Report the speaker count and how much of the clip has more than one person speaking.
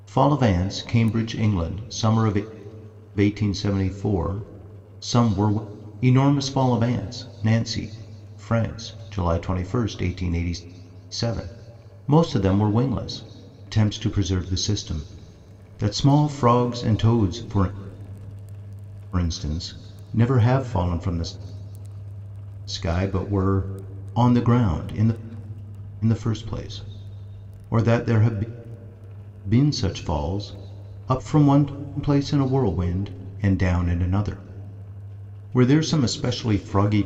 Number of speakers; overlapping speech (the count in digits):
1, no overlap